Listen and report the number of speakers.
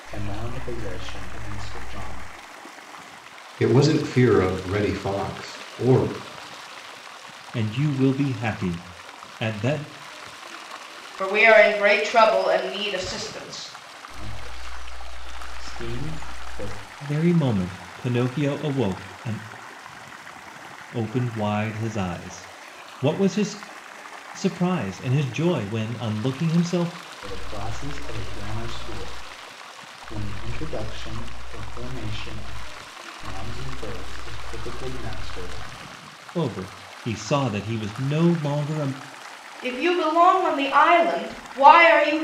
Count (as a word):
four